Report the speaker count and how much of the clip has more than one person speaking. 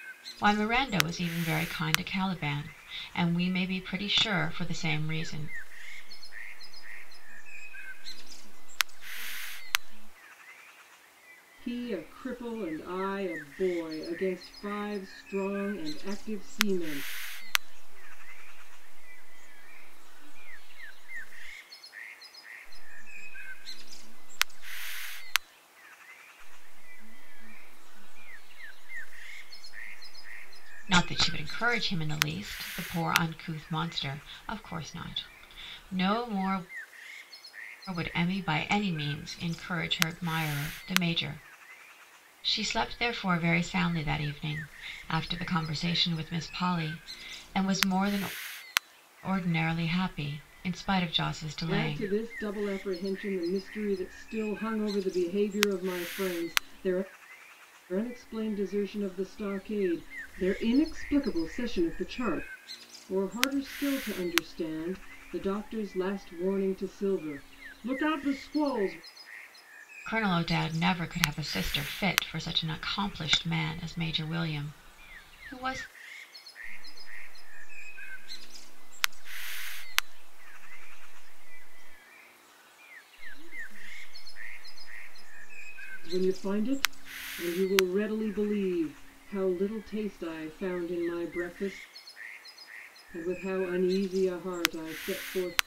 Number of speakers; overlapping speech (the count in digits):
3, about 6%